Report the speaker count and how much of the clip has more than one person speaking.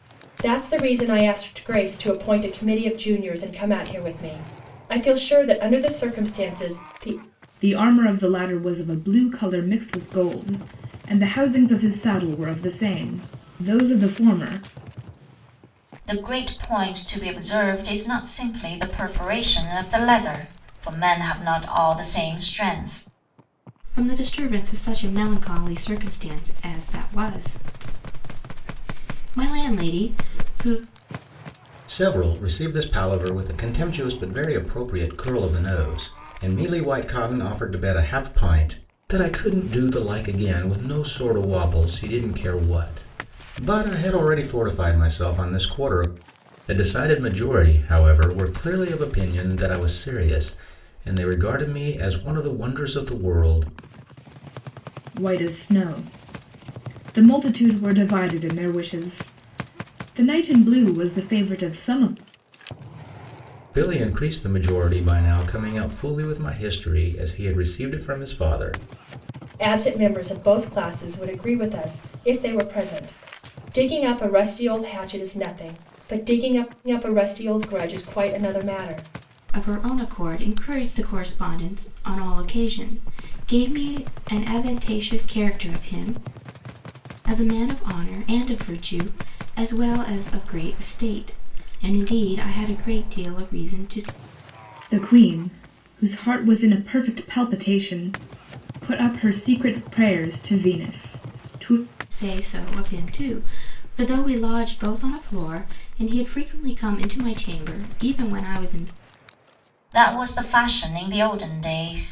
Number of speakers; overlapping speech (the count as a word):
five, no overlap